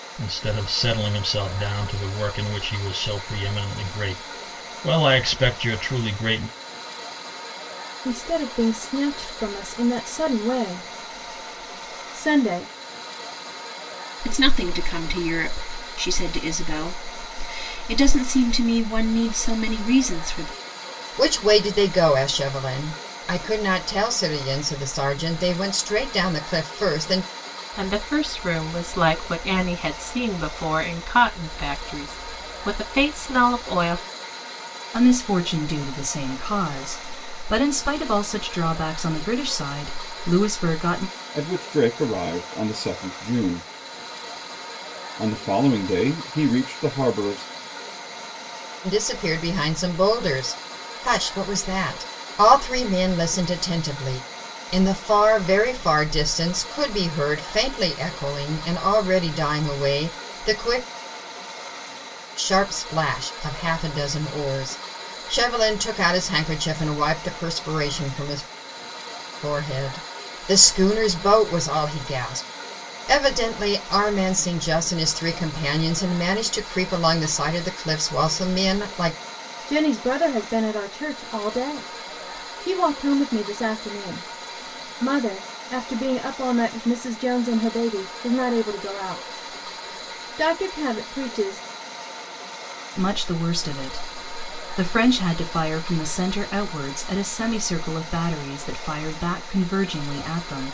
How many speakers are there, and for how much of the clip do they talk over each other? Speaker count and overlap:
7, no overlap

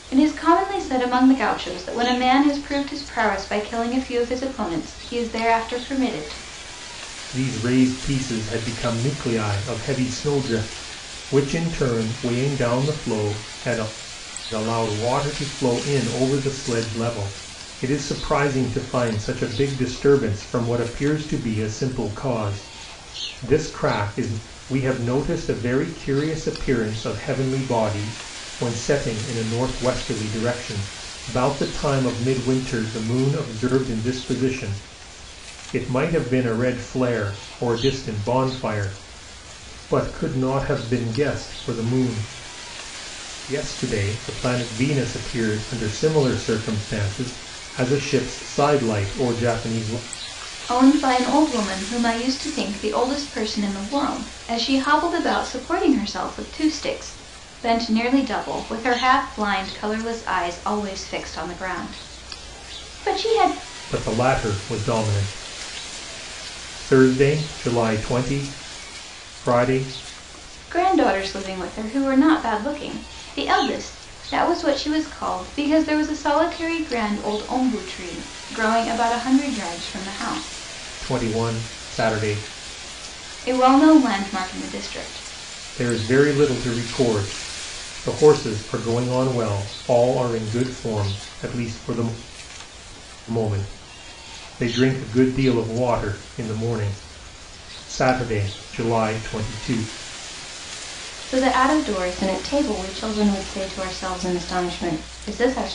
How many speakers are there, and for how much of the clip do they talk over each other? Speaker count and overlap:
2, no overlap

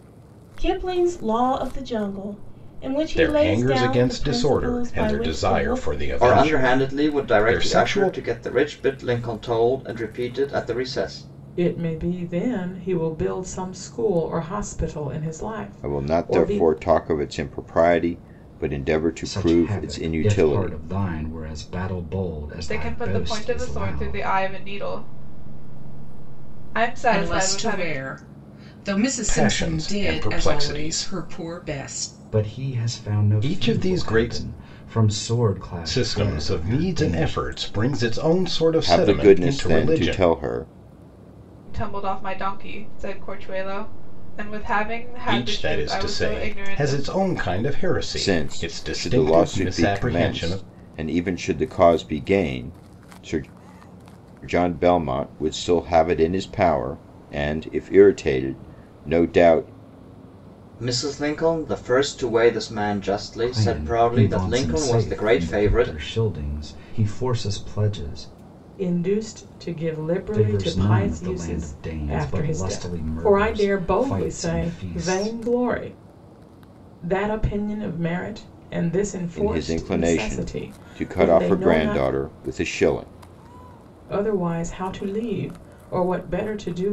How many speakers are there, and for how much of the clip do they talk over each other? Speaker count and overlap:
8, about 38%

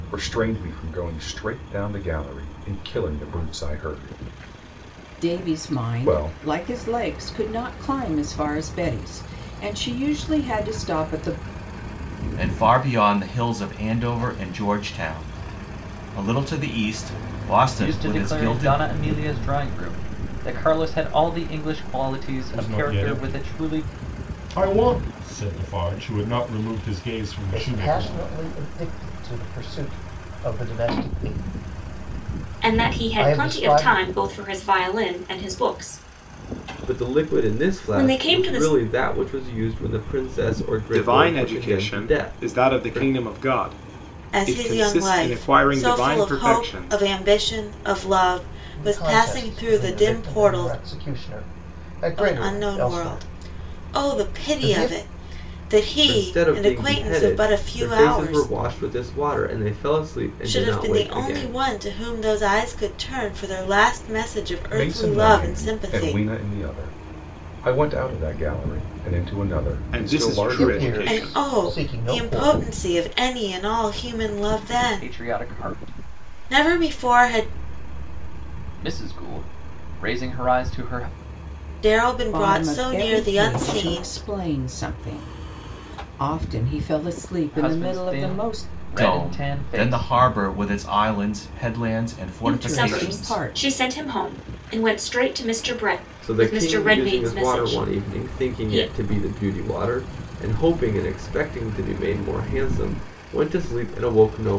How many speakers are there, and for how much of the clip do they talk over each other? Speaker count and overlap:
10, about 35%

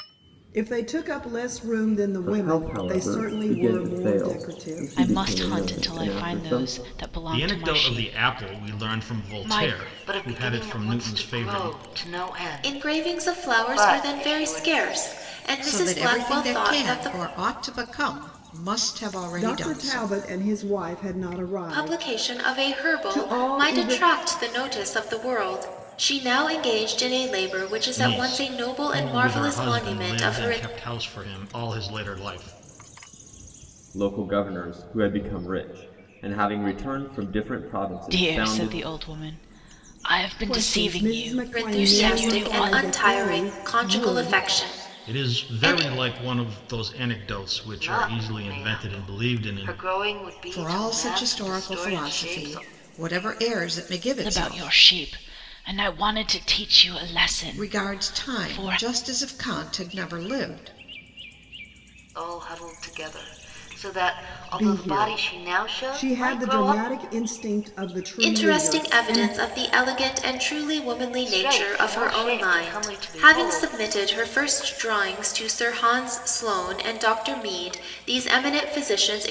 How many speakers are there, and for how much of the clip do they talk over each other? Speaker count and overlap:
7, about 45%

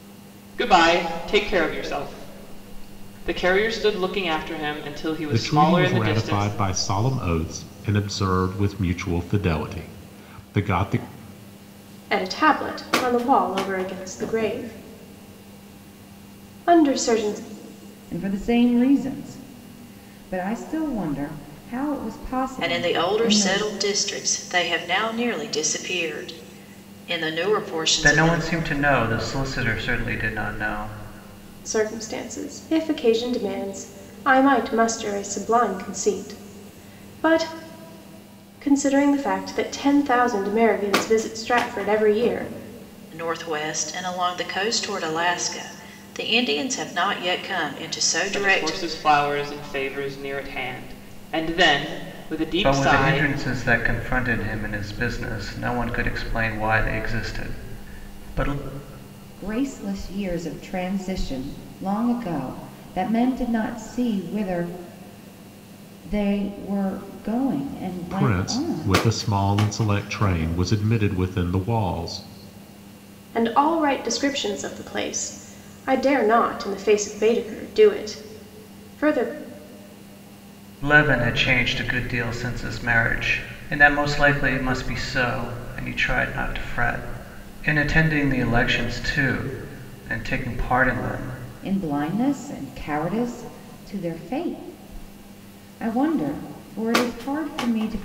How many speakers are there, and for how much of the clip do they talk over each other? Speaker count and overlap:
6, about 5%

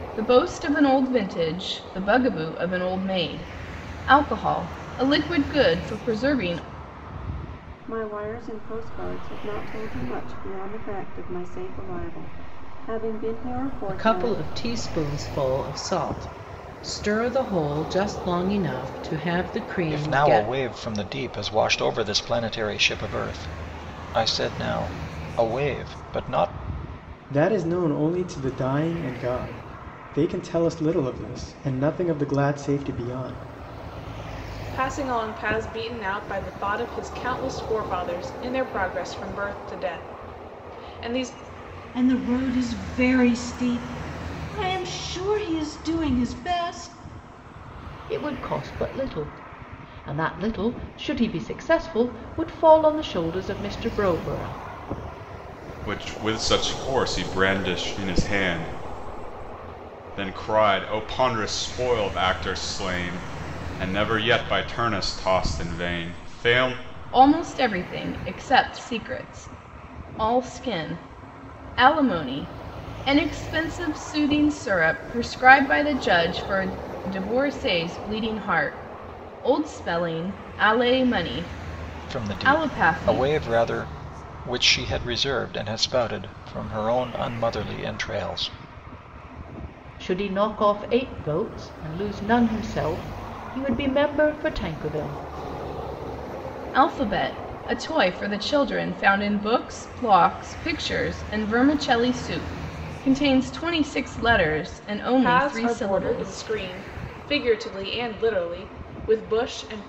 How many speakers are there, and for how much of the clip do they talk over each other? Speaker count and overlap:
9, about 4%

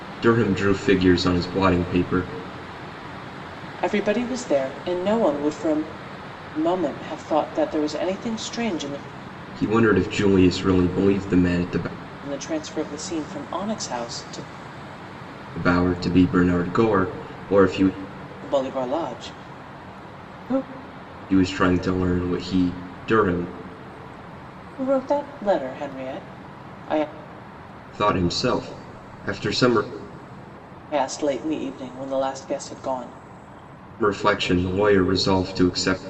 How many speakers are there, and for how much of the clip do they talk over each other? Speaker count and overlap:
2, no overlap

